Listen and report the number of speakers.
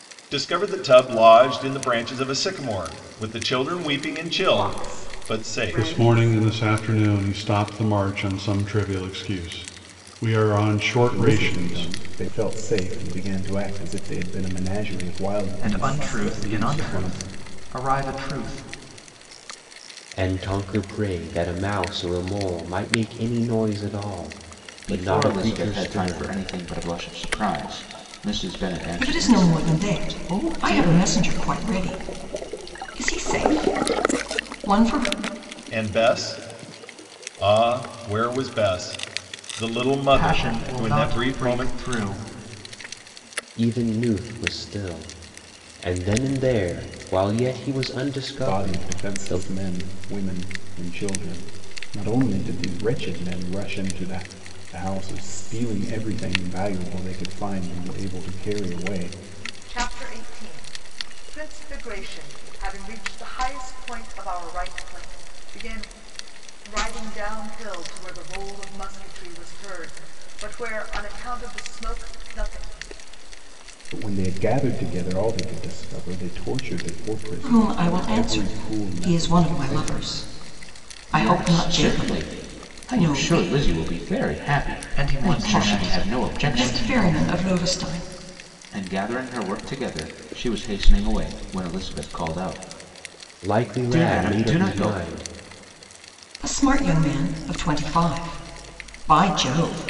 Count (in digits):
8